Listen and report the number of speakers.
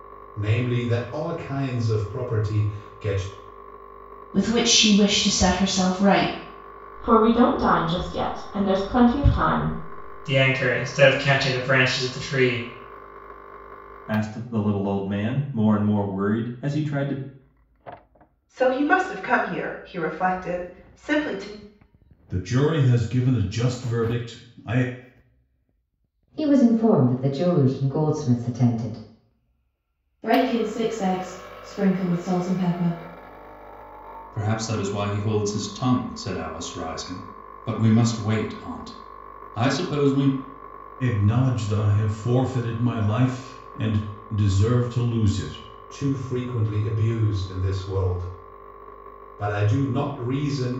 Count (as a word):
ten